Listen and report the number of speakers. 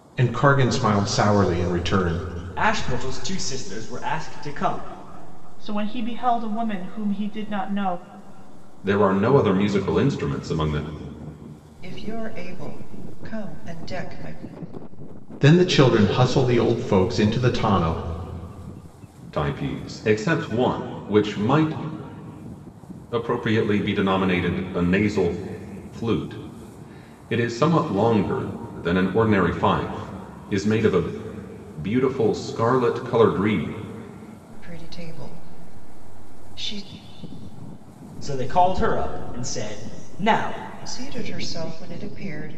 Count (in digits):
5